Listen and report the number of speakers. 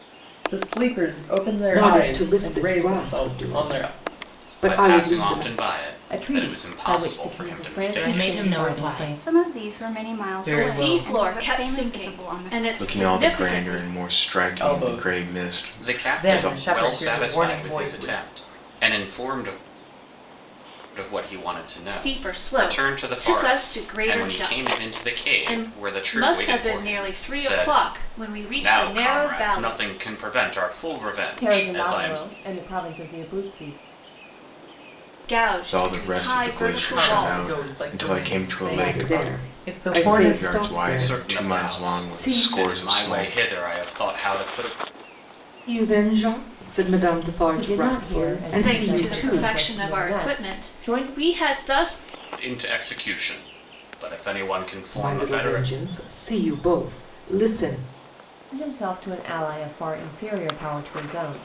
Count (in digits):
8